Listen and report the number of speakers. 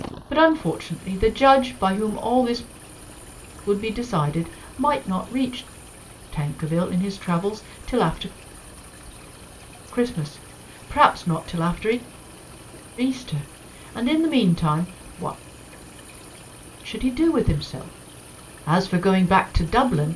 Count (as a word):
one